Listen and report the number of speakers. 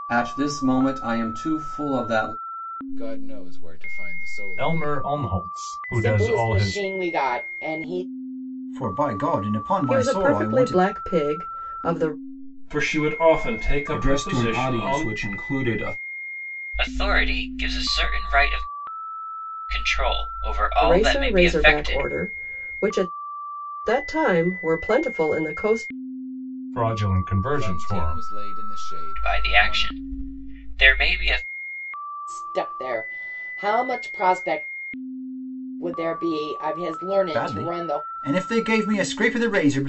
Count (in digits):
9